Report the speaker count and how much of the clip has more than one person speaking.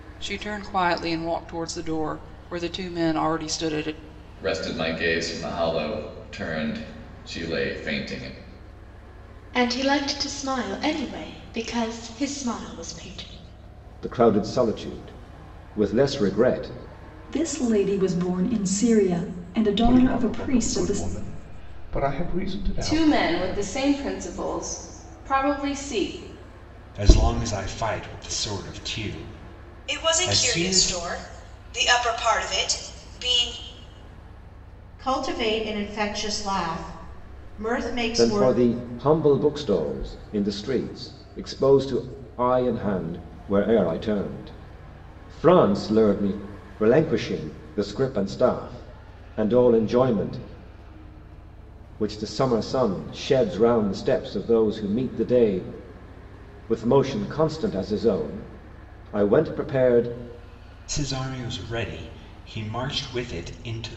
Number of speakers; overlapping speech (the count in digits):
10, about 6%